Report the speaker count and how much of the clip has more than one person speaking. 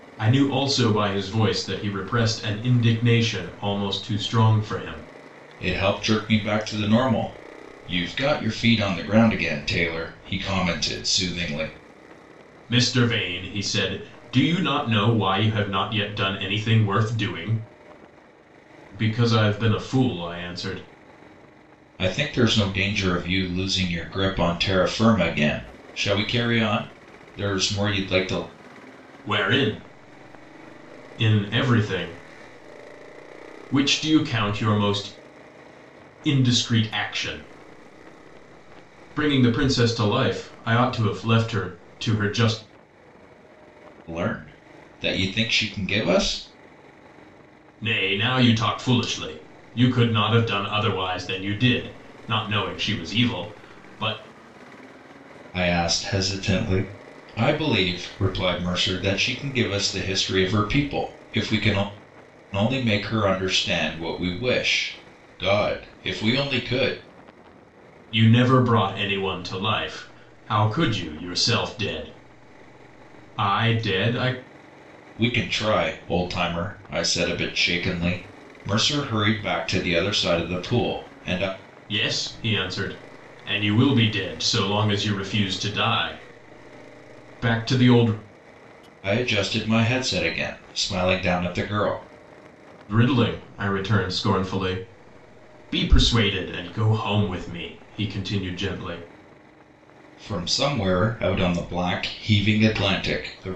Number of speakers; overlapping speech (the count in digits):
2, no overlap